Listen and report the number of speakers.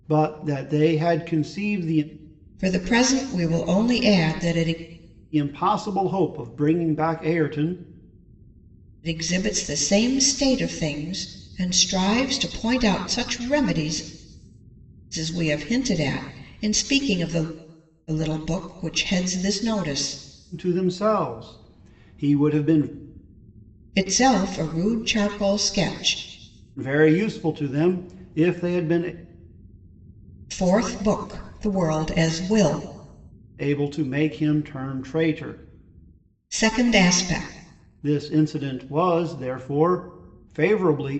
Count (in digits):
2